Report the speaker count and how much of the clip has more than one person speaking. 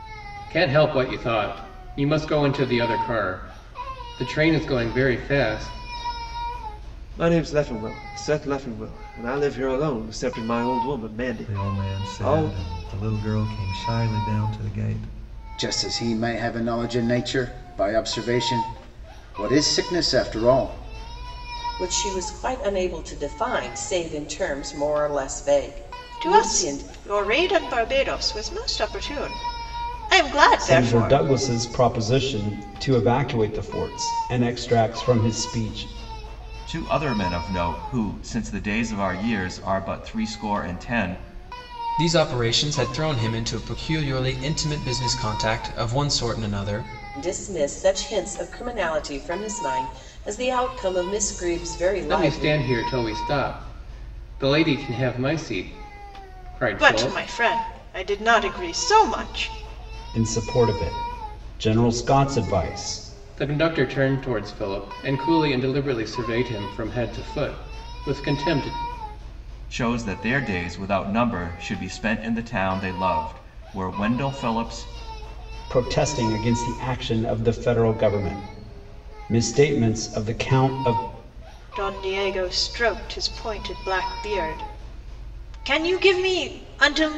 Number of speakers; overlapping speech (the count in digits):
9, about 4%